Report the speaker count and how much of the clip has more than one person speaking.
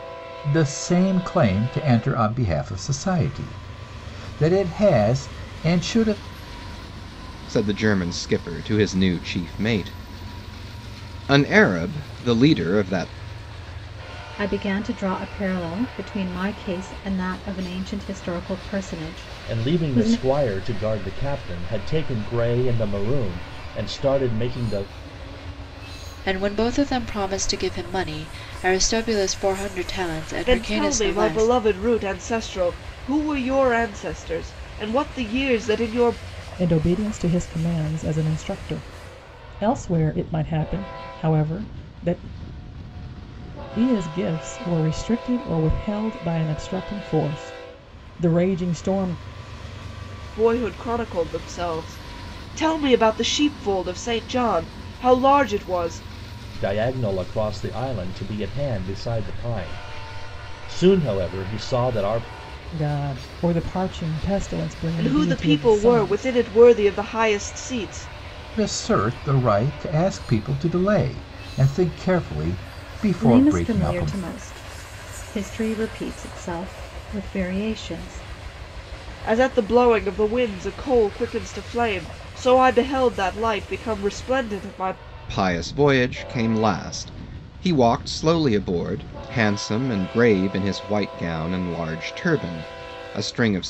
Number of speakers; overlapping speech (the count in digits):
7, about 4%